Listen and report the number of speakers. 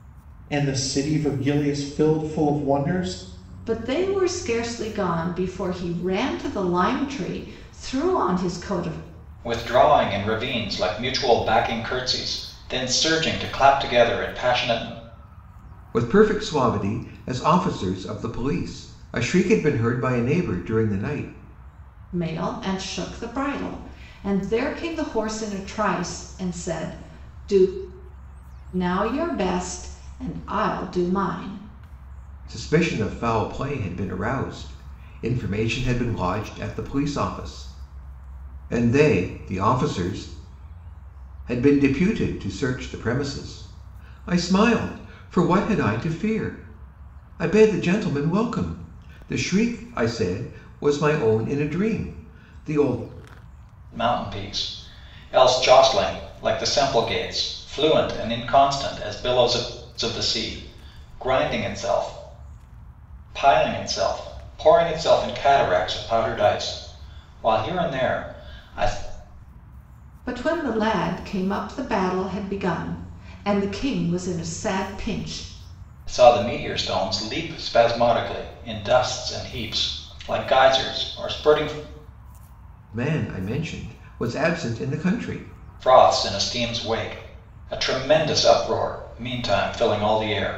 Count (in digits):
4